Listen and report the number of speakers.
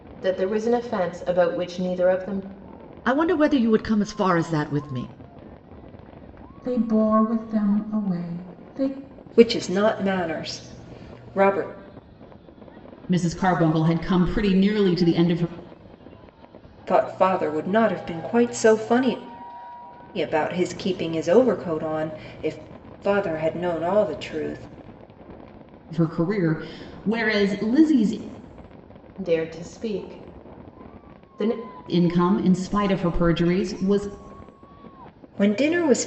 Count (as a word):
five